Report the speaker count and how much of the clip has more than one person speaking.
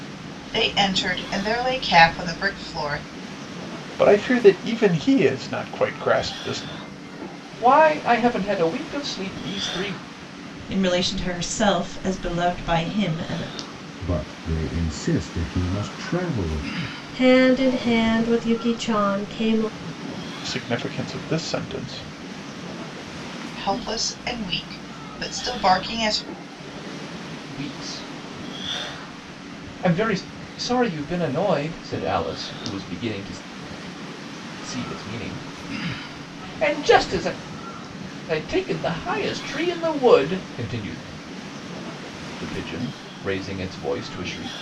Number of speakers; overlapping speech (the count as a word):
six, no overlap